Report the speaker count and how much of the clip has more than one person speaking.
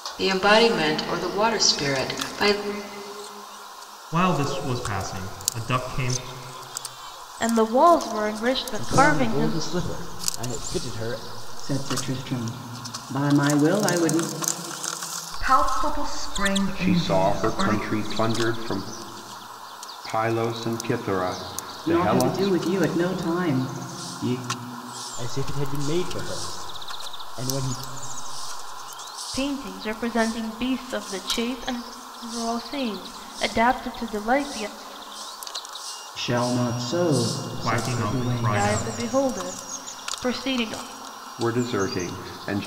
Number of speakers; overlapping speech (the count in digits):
7, about 10%